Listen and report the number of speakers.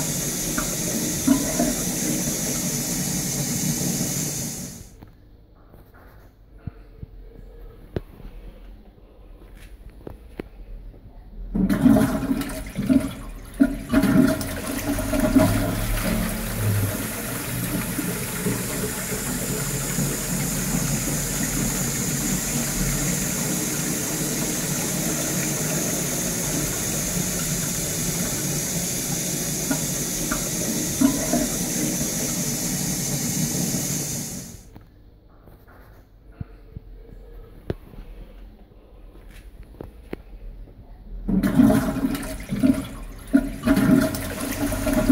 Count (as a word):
zero